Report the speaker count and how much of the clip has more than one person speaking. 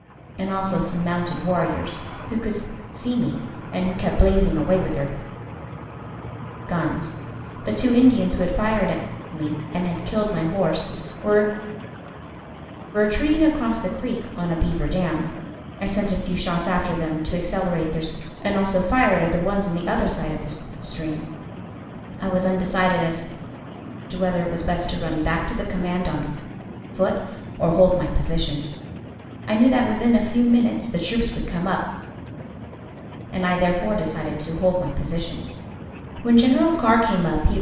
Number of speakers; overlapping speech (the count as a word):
one, no overlap